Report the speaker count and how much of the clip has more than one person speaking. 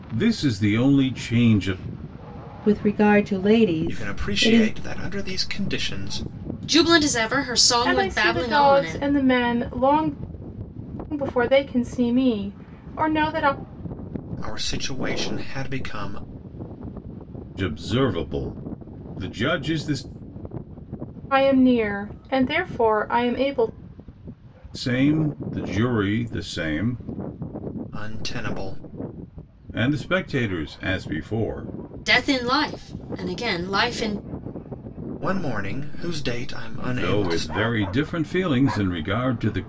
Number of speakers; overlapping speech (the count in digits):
5, about 7%